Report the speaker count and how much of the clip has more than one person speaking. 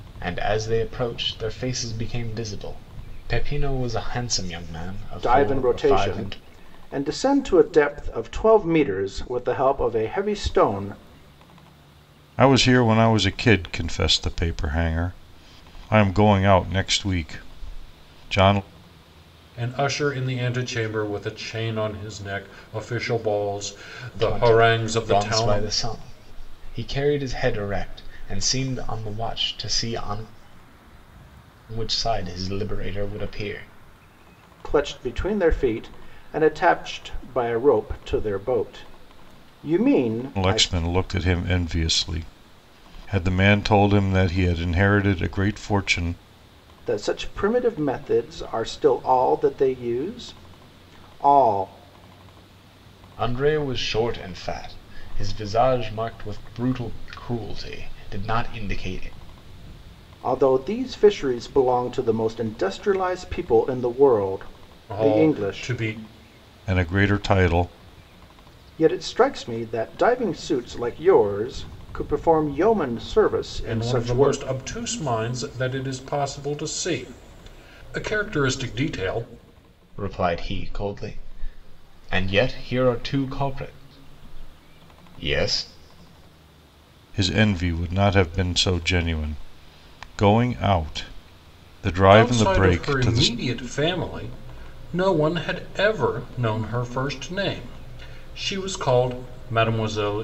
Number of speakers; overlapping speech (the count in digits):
4, about 6%